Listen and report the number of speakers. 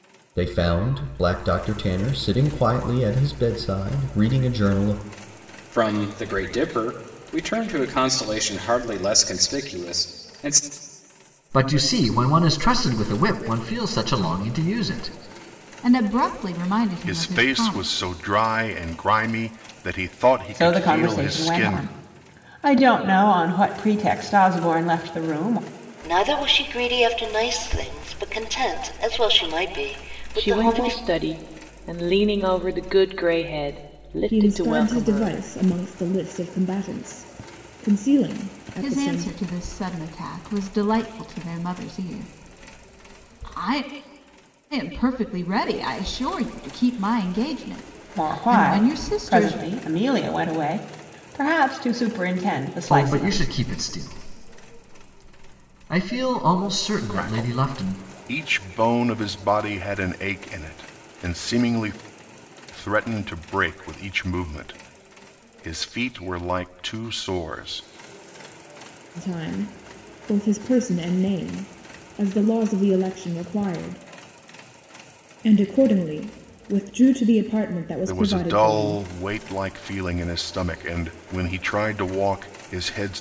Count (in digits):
9